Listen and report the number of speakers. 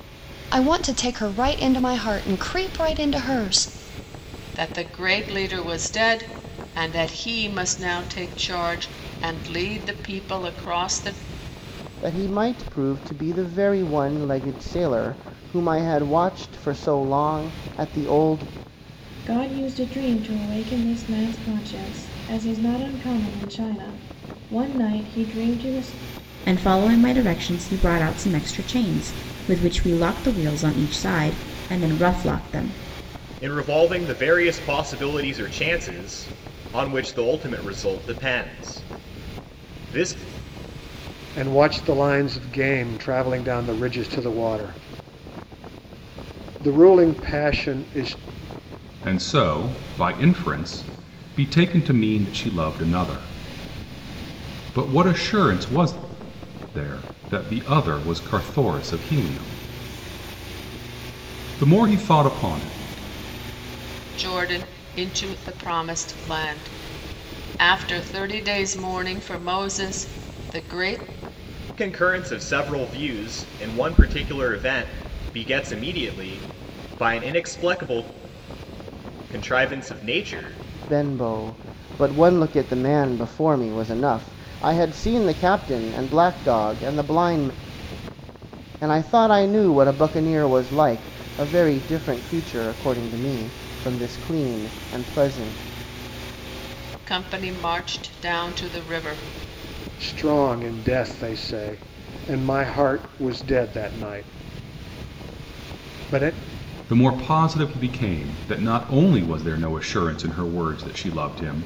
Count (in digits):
8